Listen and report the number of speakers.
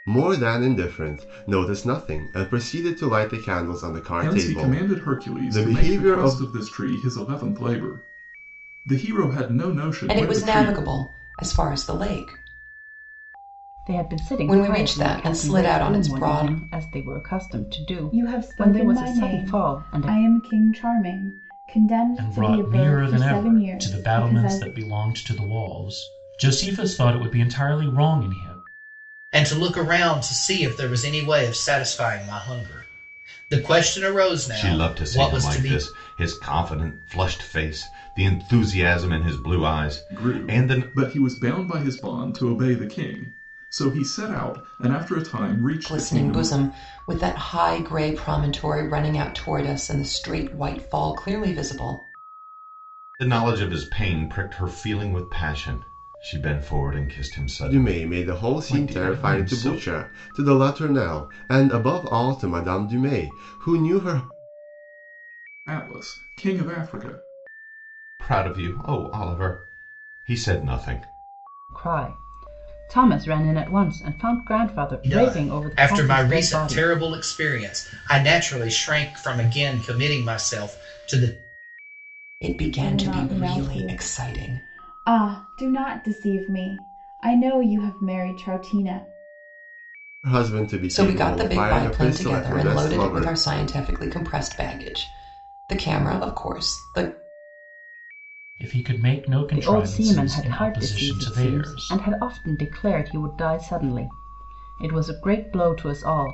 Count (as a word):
eight